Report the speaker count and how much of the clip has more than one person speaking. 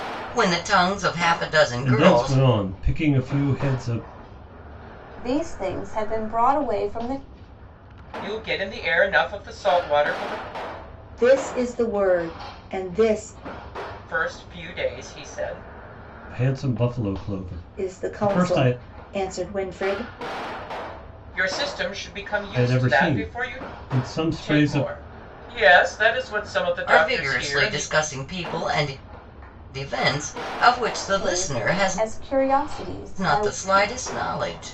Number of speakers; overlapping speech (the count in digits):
5, about 16%